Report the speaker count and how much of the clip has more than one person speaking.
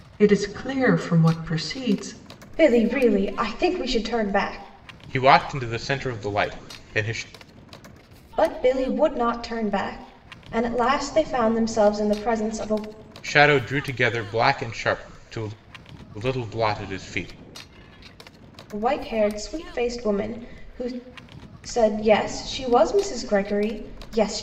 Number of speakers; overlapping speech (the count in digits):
3, no overlap